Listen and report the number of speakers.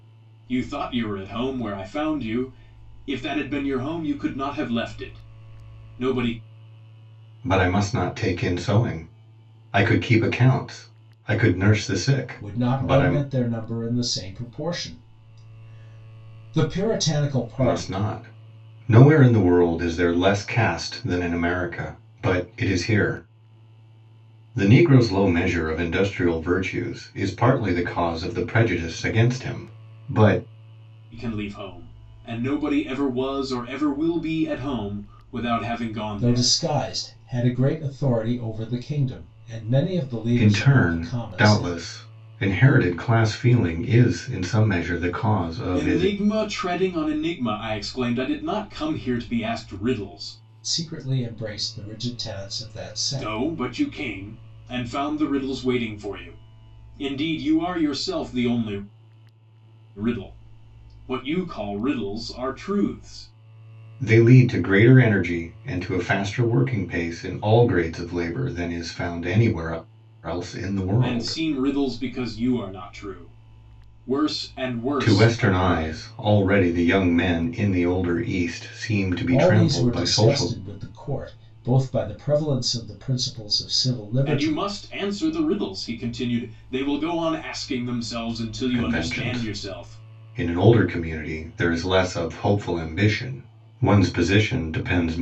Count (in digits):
3